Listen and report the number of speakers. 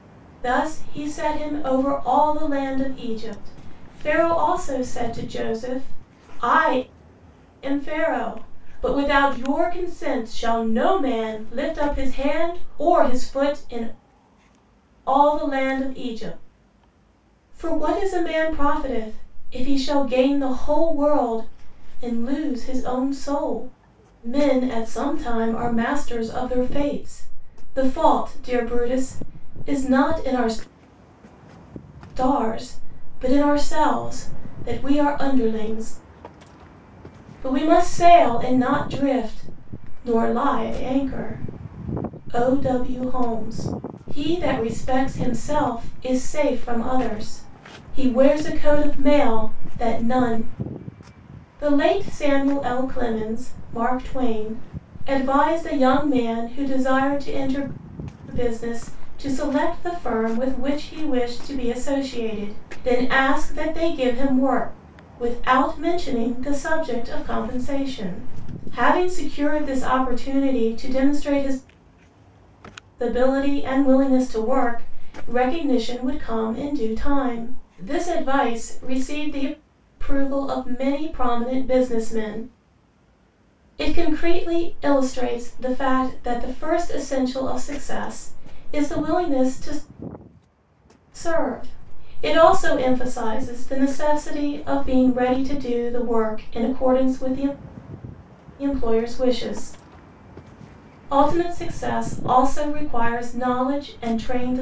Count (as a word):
one